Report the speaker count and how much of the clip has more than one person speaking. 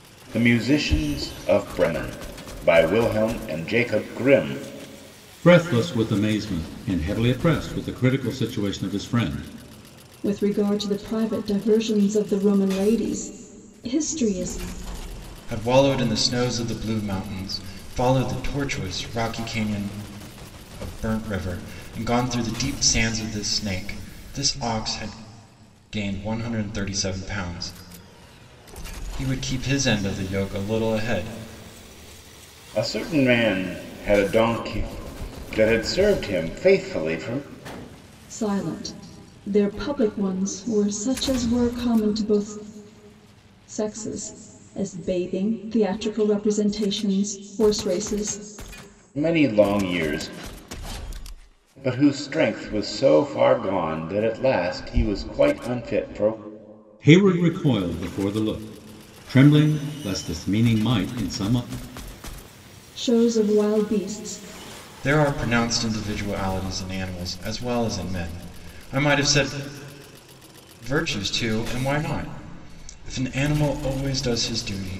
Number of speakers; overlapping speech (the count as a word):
four, no overlap